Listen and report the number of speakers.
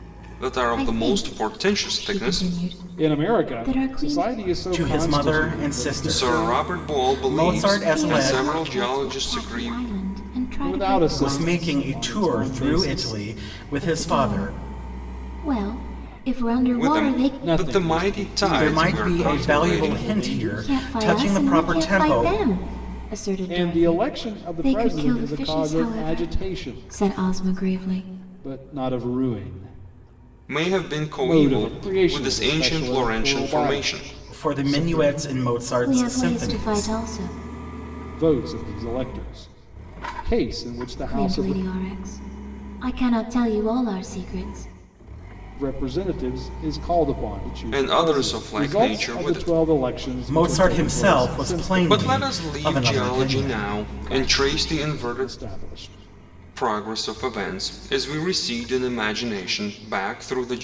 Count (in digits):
4